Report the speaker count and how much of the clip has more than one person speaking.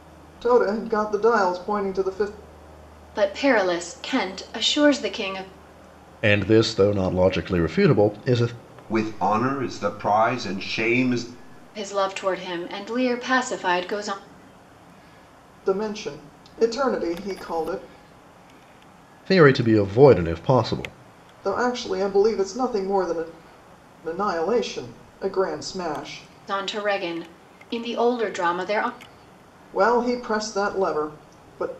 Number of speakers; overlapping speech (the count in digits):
4, no overlap